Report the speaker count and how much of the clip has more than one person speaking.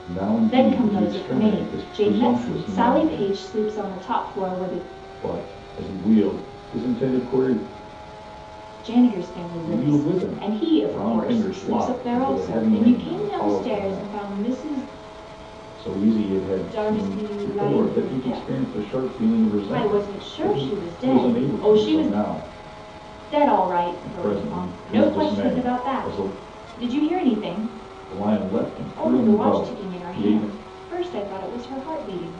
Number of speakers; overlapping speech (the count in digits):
2, about 48%